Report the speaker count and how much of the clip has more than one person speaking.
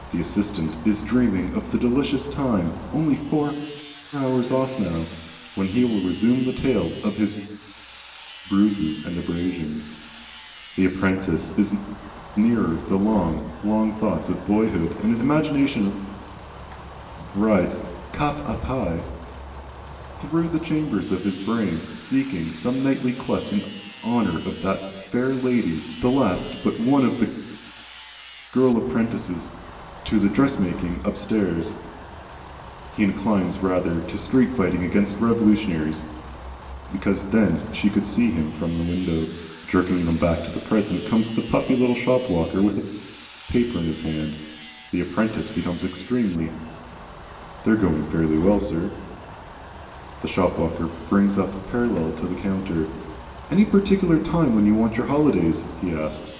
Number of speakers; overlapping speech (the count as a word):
one, no overlap